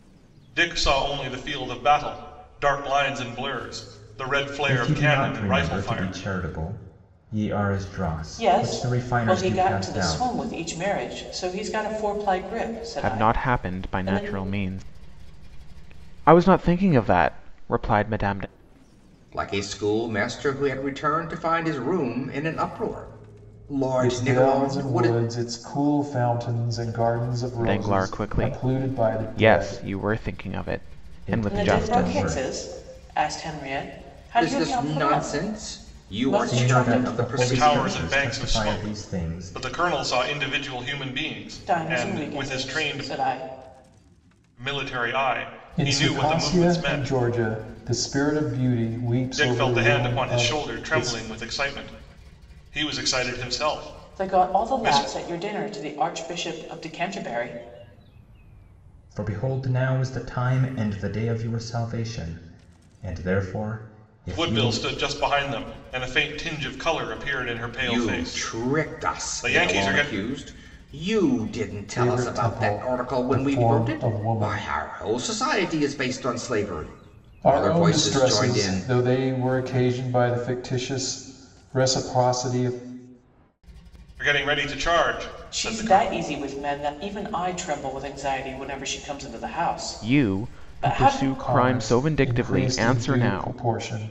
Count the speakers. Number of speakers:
six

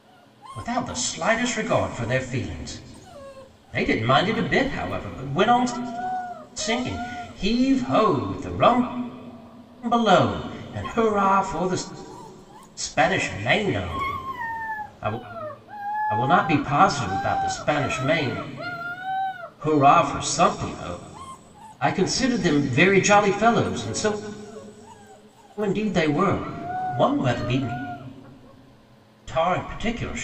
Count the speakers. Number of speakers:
one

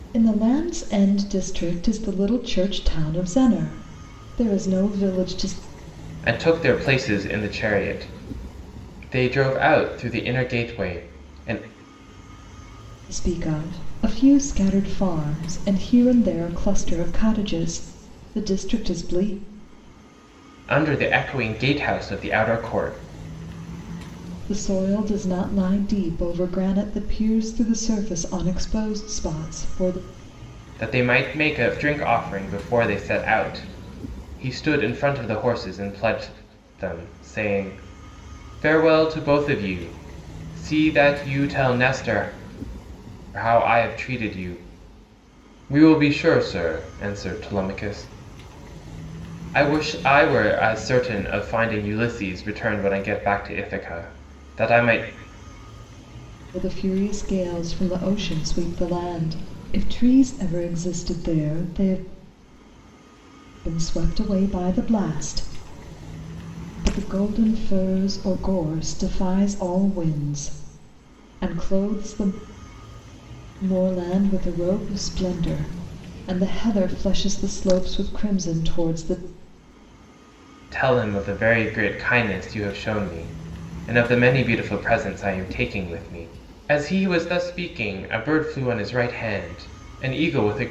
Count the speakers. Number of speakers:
two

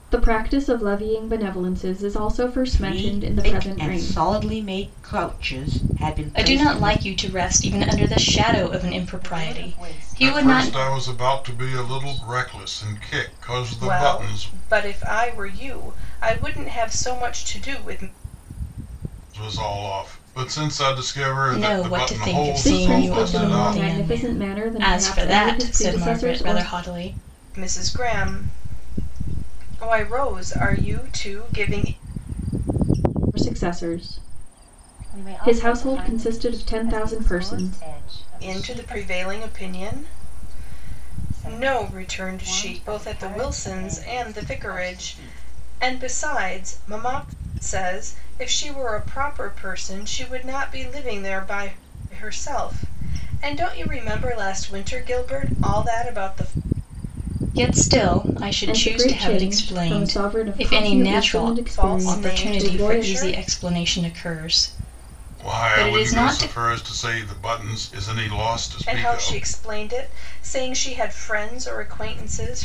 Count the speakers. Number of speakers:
six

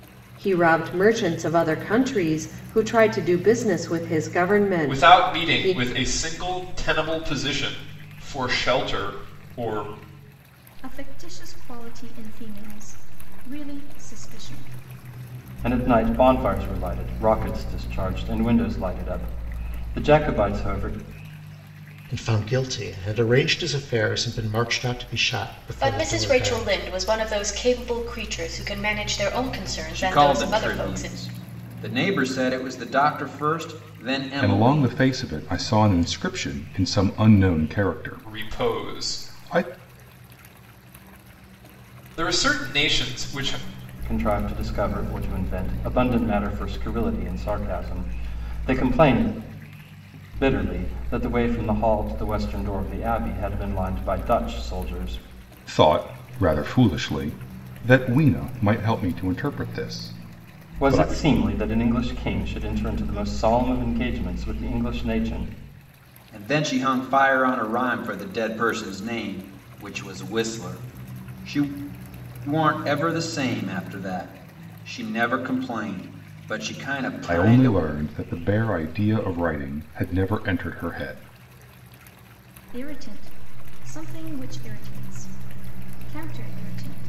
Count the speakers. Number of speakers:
eight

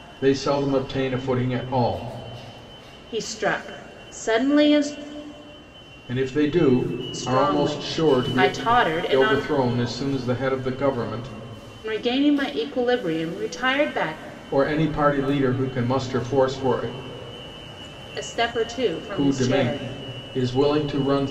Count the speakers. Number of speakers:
two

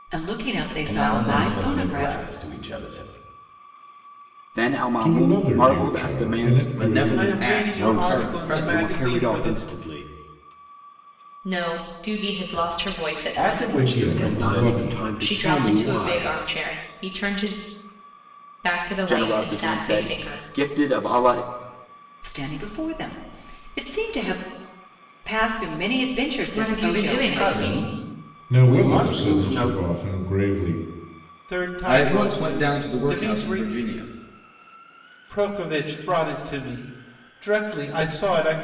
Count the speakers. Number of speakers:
eight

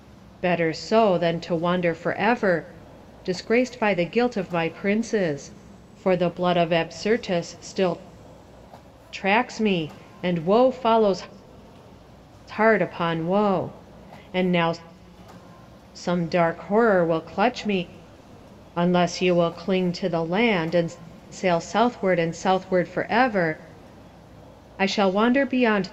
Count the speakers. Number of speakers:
one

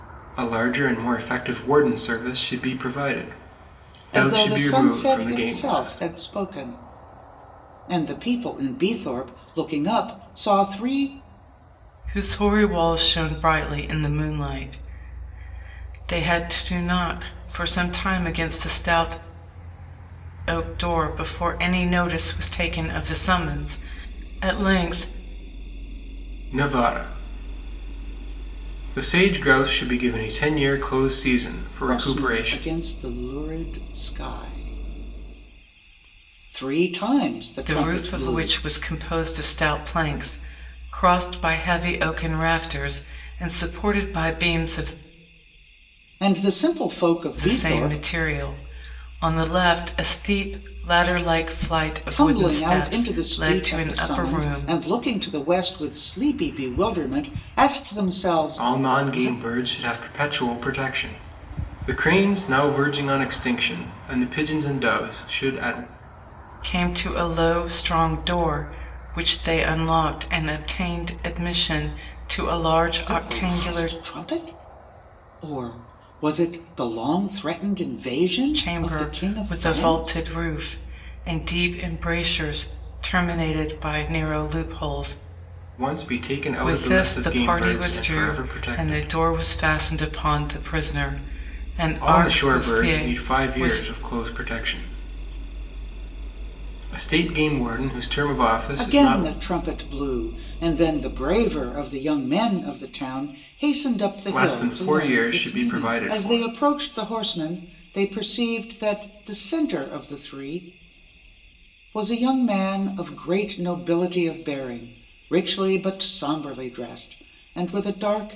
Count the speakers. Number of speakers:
three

